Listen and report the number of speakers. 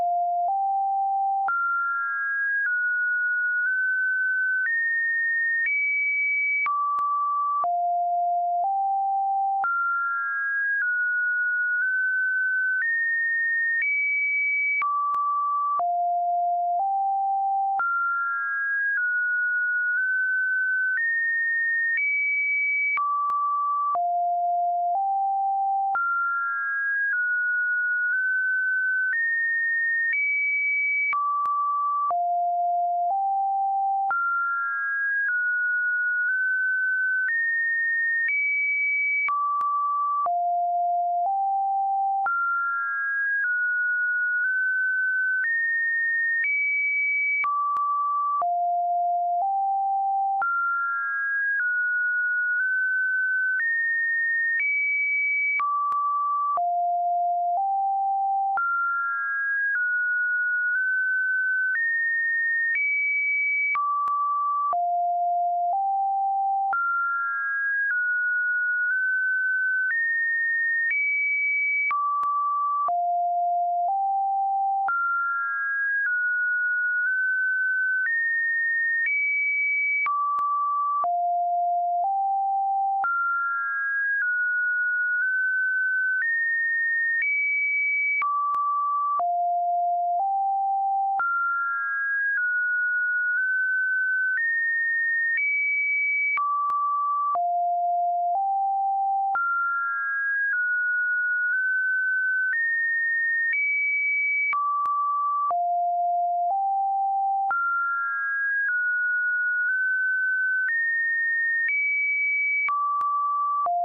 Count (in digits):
0